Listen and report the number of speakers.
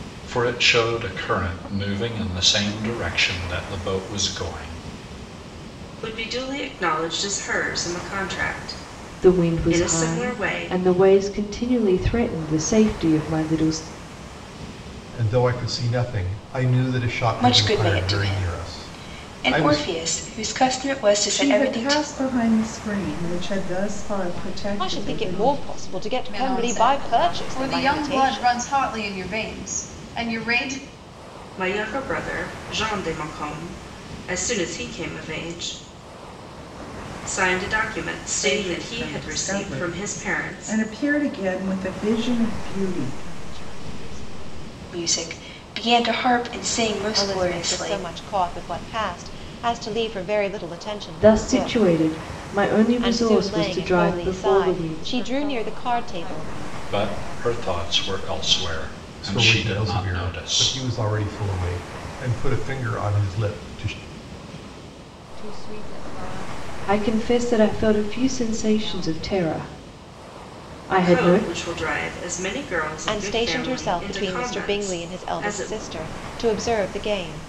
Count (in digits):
9